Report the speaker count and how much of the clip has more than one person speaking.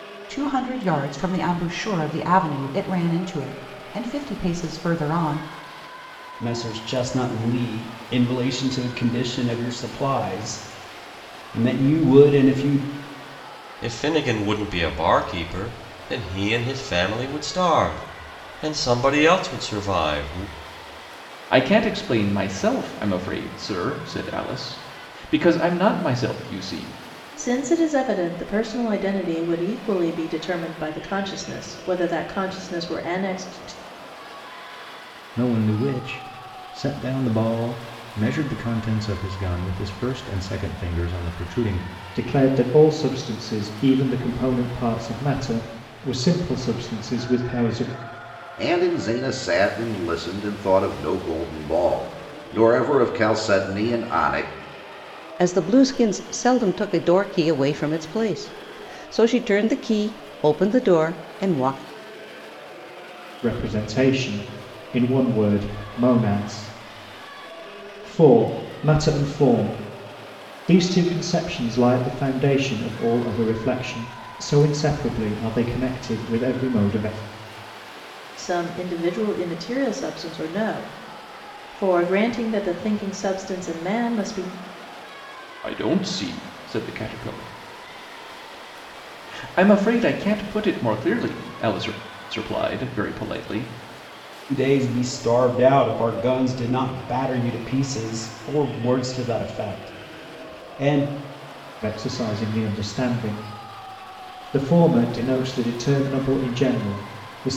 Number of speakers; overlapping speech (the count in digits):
9, no overlap